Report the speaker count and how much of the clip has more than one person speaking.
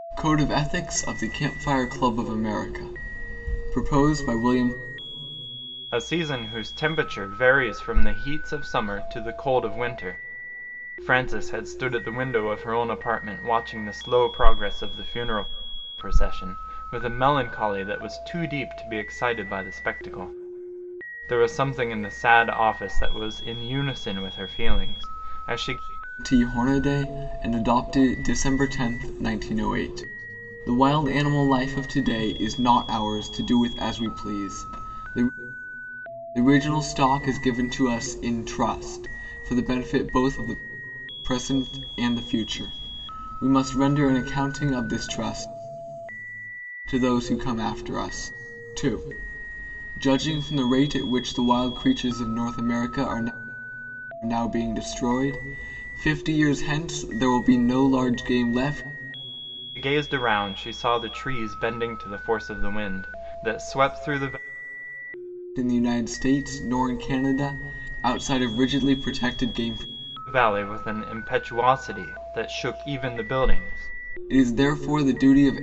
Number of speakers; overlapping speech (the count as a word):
two, no overlap